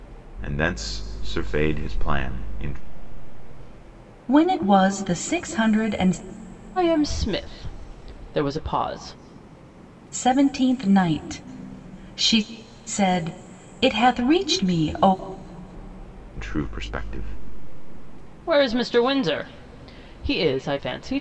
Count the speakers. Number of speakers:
three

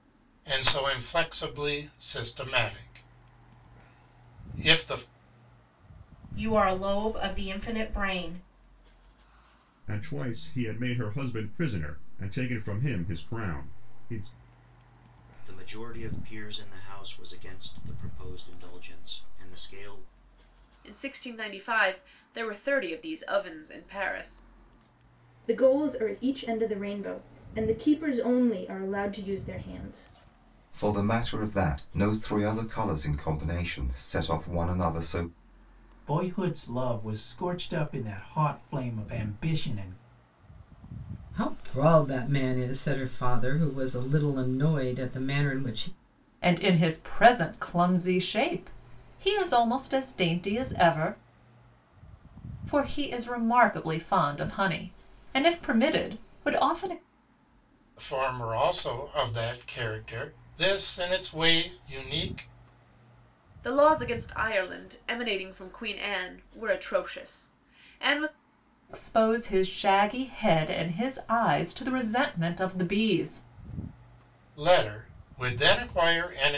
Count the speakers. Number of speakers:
ten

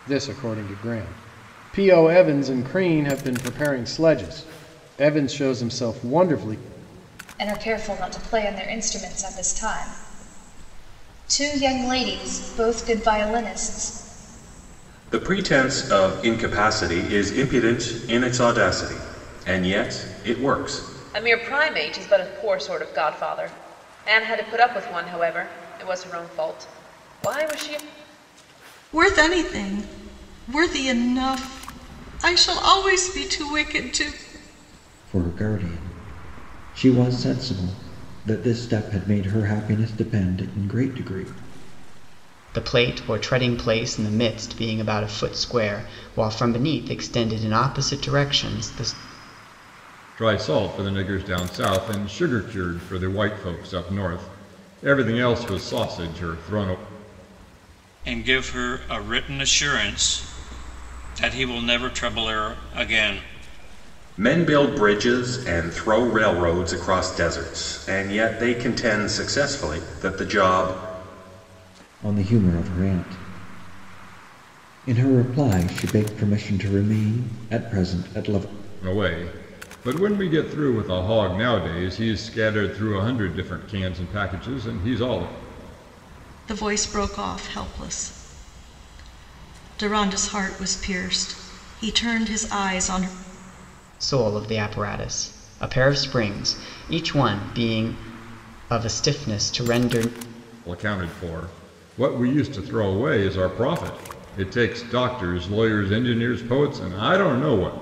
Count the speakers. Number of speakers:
nine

